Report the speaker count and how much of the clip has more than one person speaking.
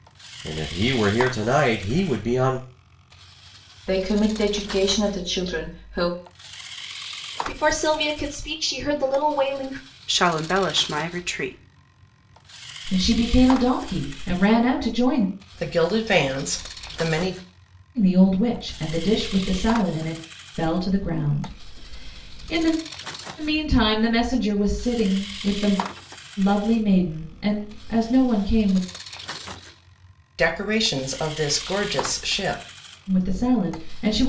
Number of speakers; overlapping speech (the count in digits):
6, no overlap